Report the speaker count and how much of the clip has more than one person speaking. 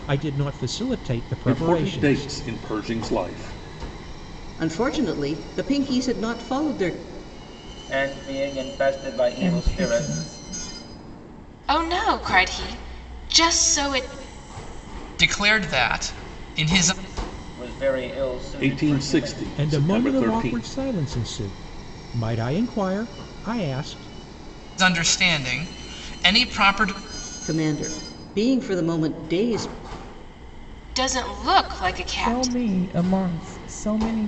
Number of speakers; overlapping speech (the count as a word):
seven, about 12%